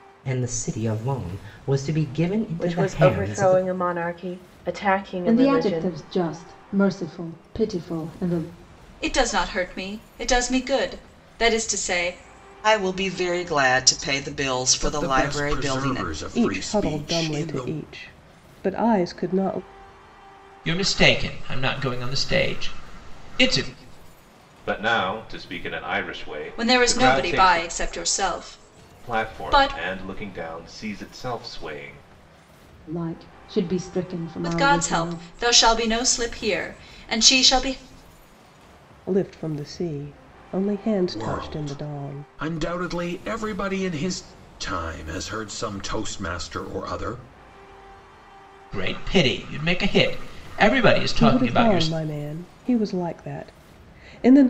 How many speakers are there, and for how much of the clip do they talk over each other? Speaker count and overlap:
9, about 17%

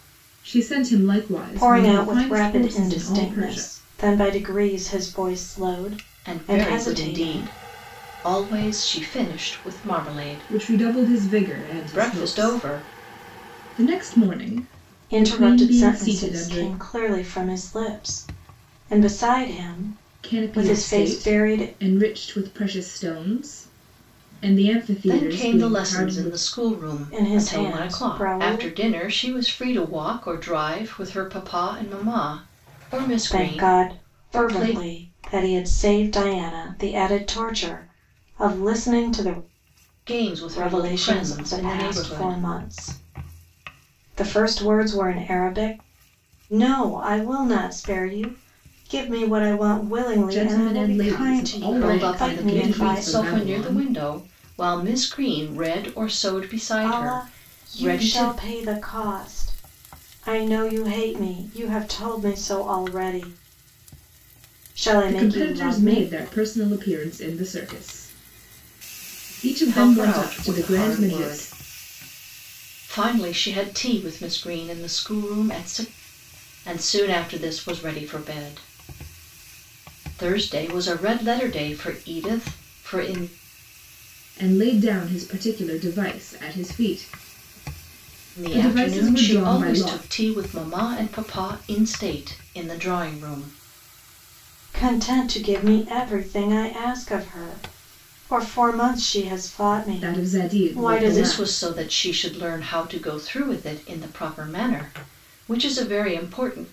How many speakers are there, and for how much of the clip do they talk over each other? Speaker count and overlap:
3, about 25%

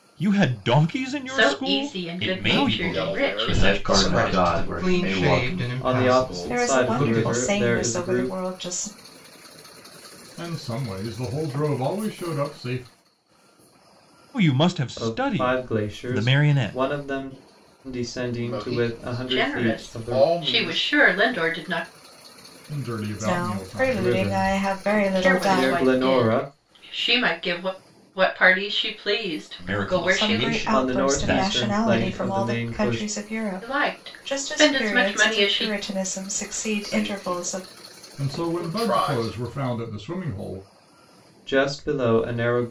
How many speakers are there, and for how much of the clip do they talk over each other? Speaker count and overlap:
9, about 53%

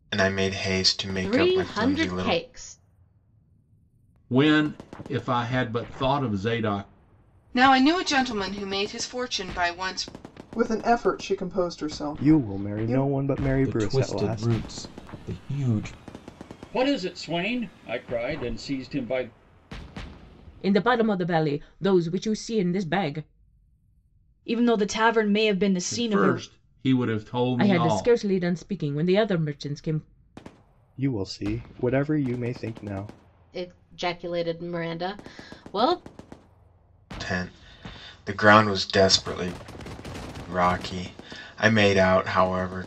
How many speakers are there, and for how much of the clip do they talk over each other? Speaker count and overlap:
10, about 10%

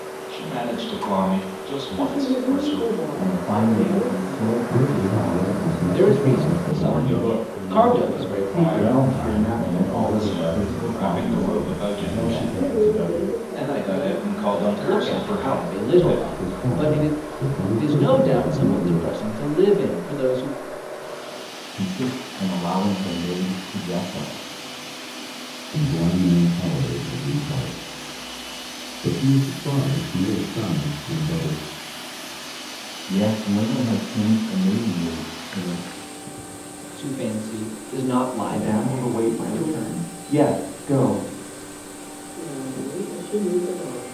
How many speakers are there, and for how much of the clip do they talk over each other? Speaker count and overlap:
8, about 40%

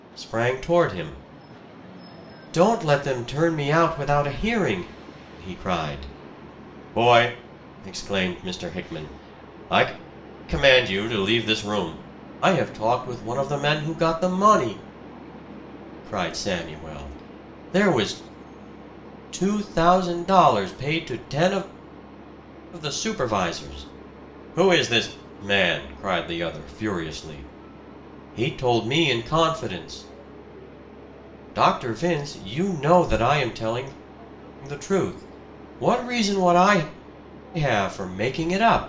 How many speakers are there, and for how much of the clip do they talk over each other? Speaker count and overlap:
1, no overlap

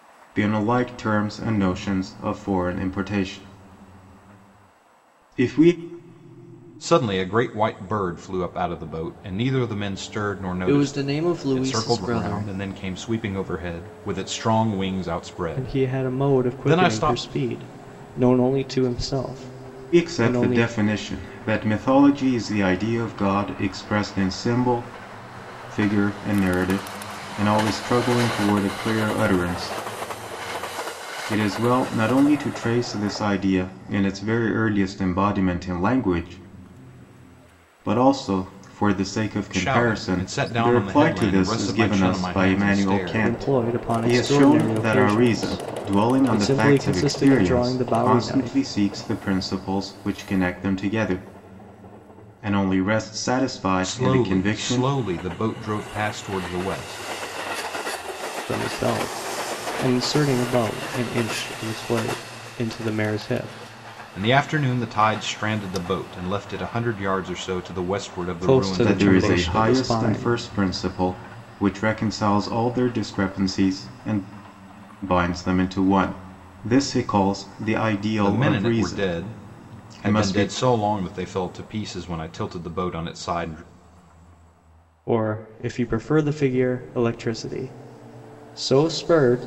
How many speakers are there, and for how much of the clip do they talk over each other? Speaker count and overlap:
3, about 21%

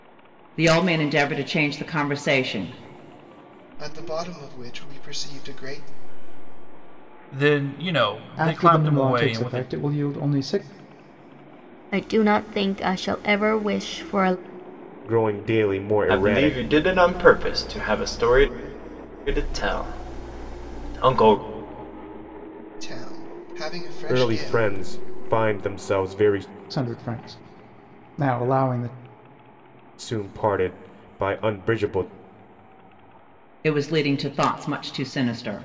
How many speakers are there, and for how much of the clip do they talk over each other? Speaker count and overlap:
7, about 7%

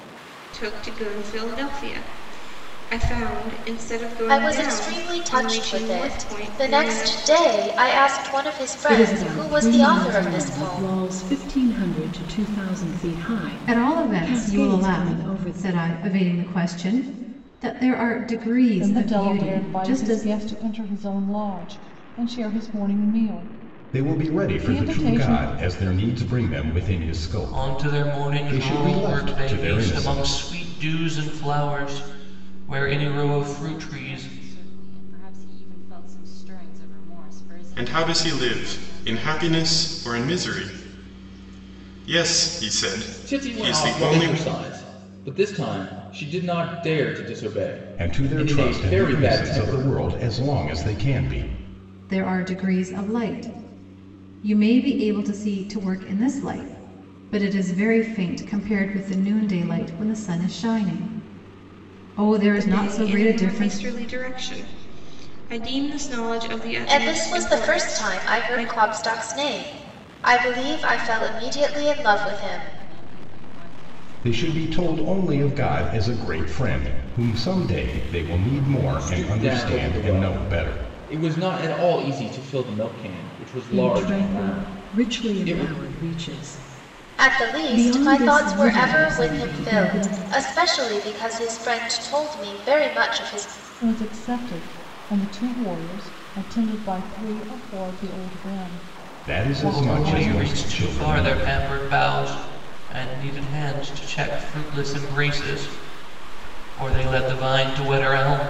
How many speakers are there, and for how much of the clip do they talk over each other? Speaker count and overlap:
10, about 34%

